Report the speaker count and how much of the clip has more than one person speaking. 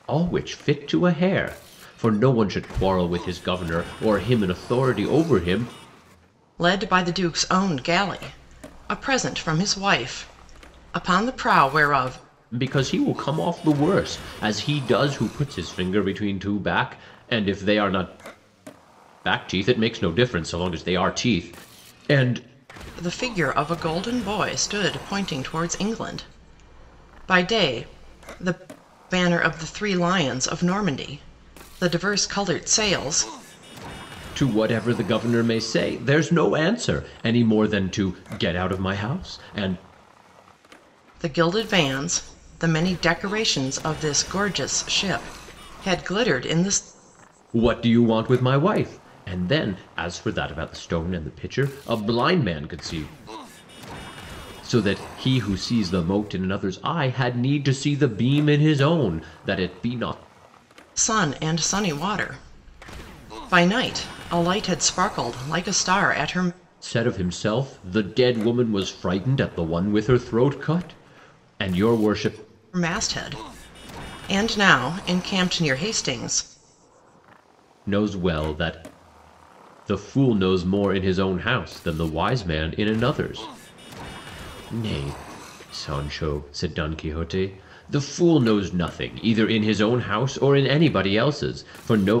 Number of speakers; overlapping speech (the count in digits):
2, no overlap